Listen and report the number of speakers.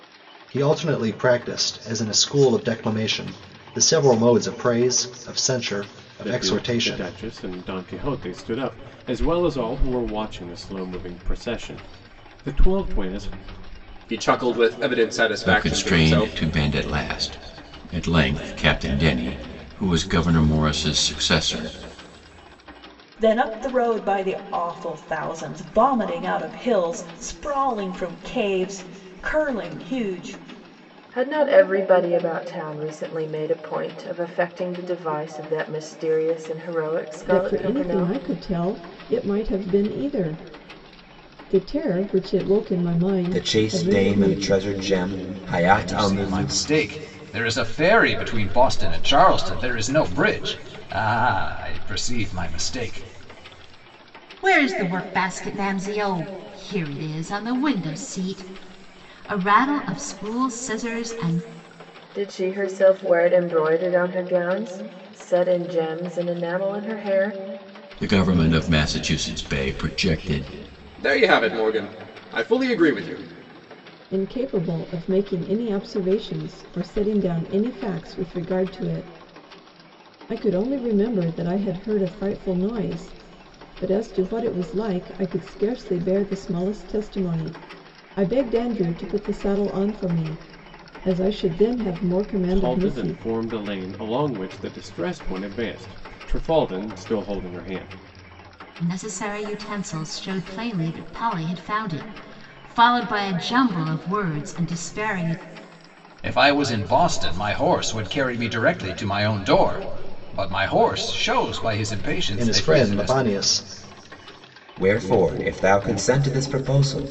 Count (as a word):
ten